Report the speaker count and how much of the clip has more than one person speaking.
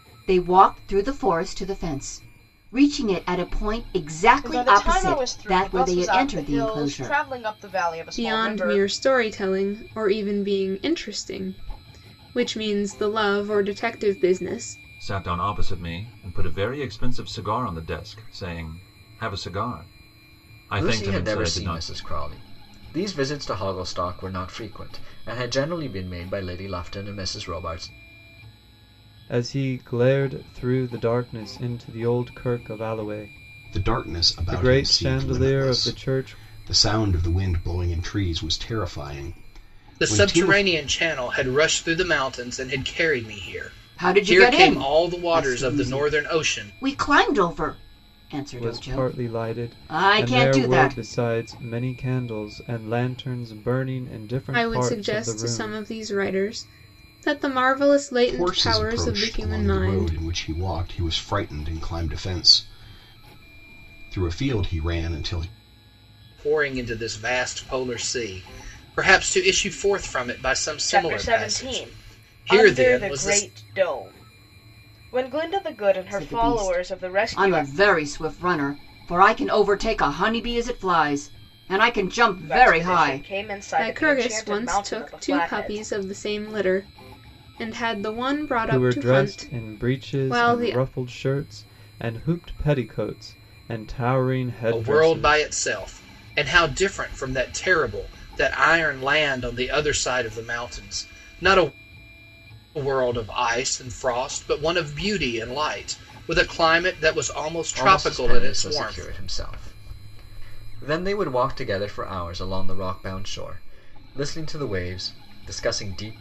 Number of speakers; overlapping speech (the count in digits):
8, about 24%